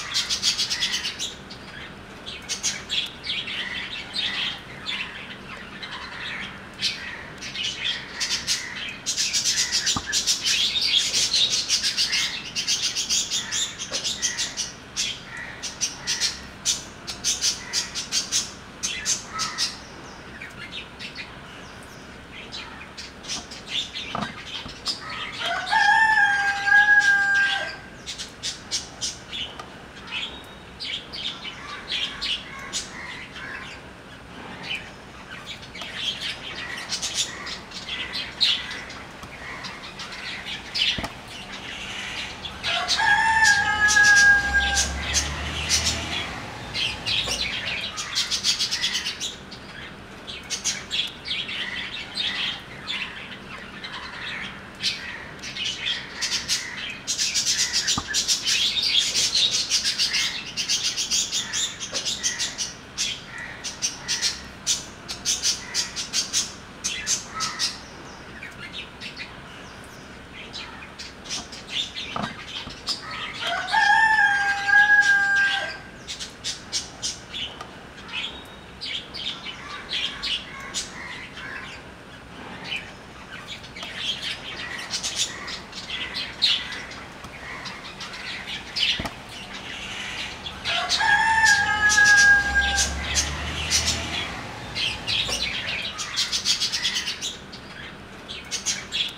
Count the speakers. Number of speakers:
zero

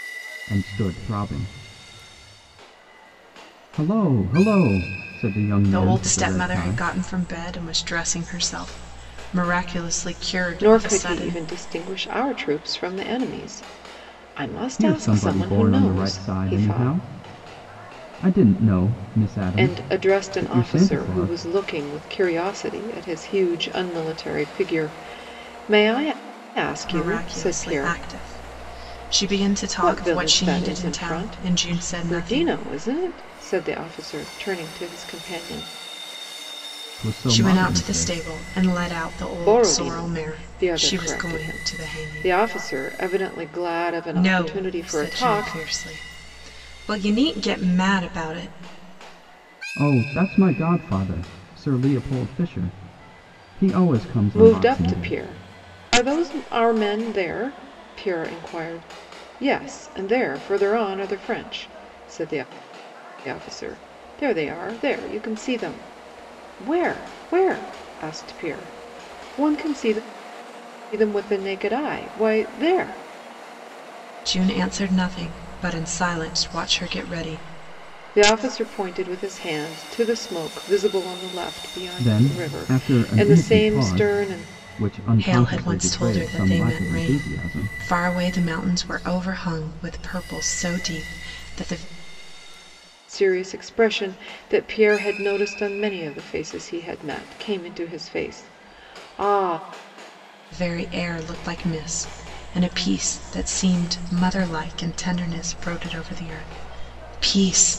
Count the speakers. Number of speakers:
three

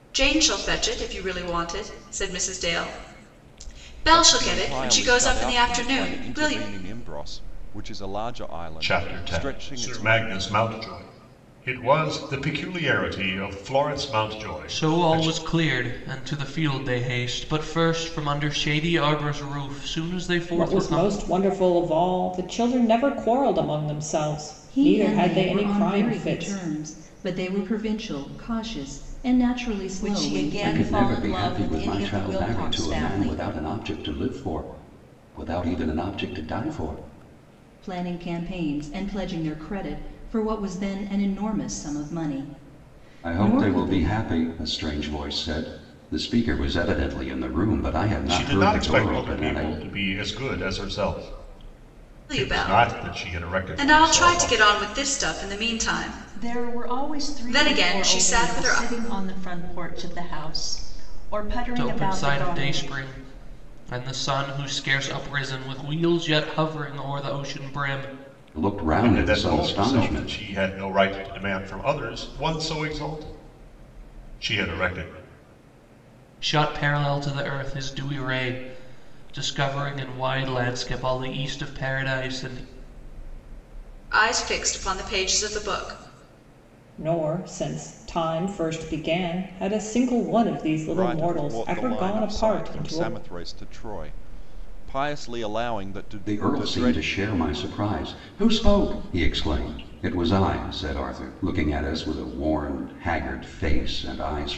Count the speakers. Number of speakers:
eight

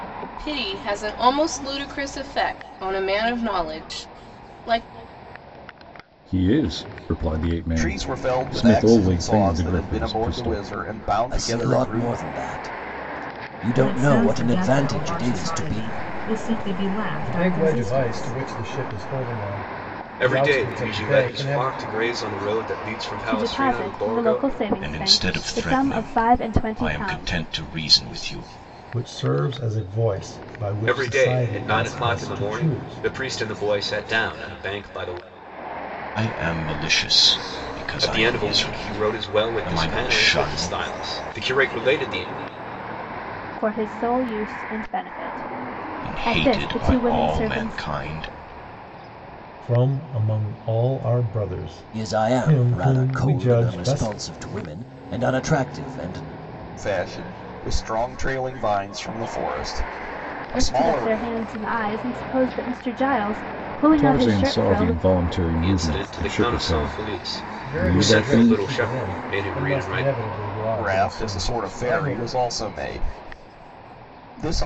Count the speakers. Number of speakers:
ten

